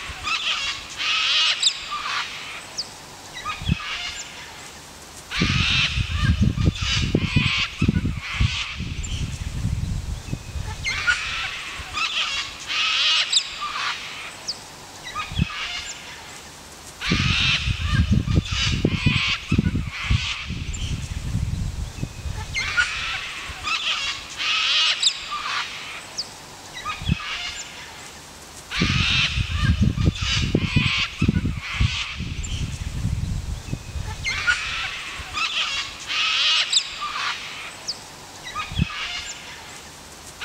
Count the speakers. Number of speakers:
0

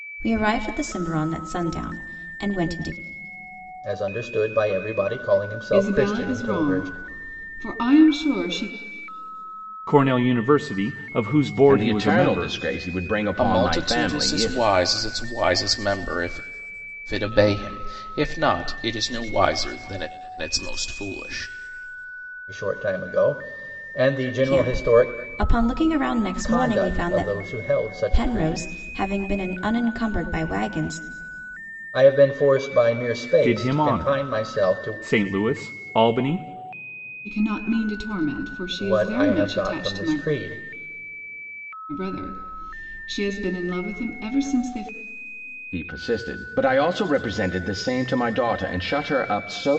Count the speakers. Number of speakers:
6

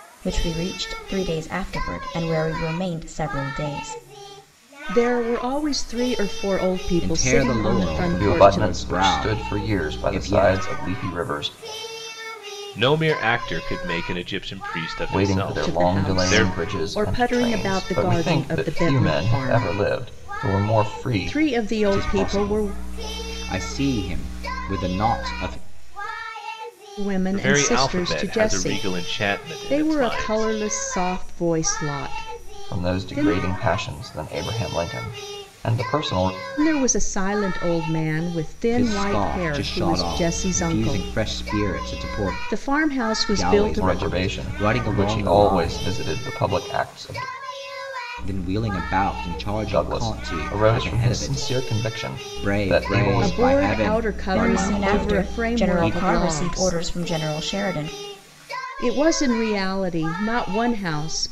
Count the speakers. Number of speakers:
5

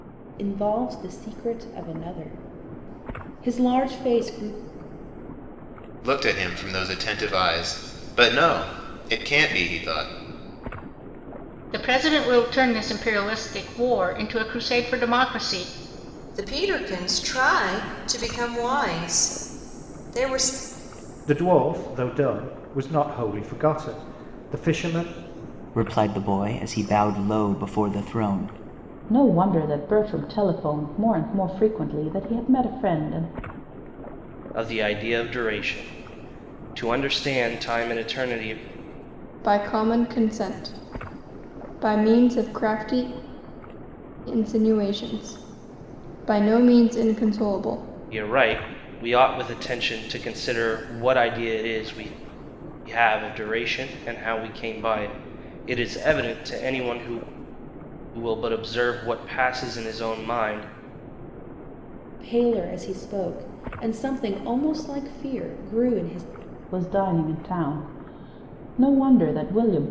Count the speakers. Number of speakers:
9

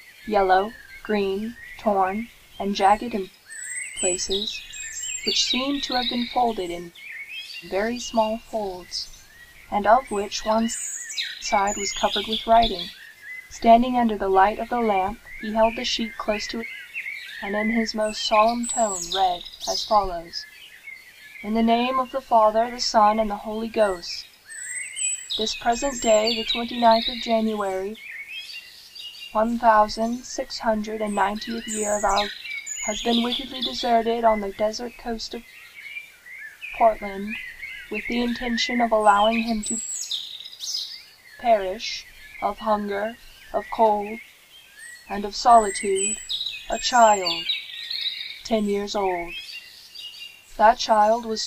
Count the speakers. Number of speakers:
1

